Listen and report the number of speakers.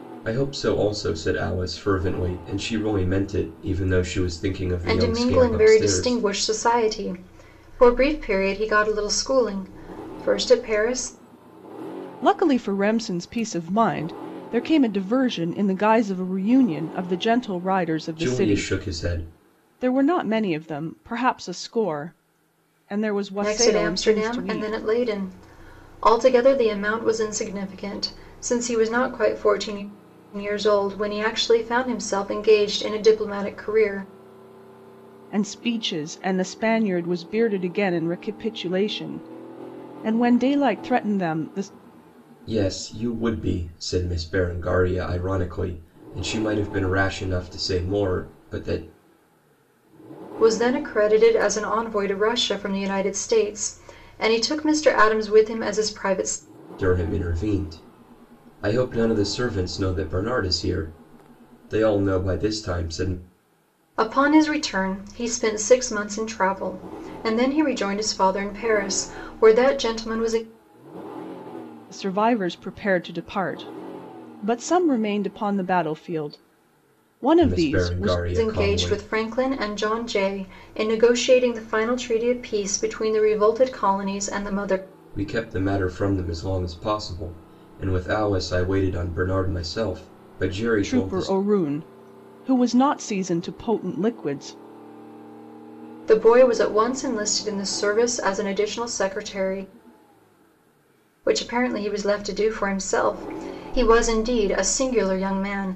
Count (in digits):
3